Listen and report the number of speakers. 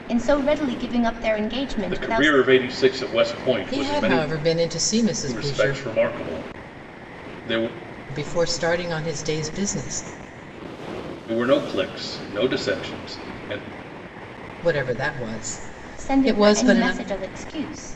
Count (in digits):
3